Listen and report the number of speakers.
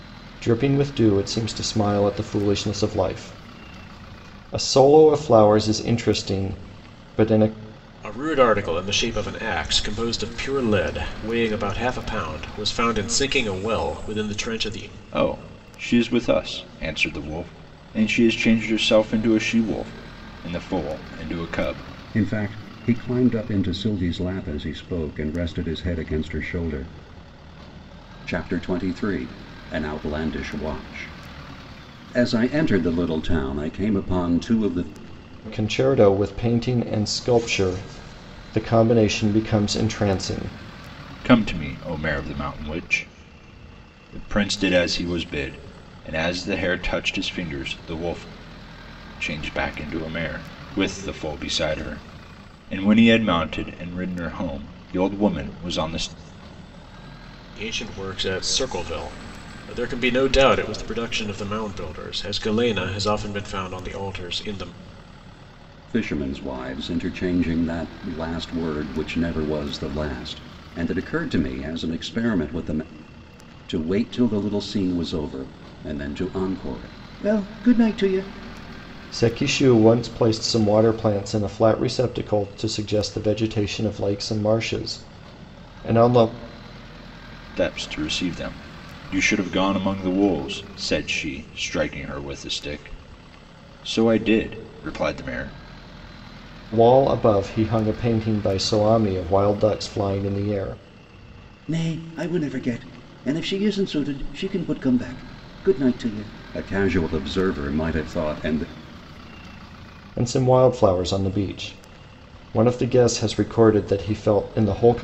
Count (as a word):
four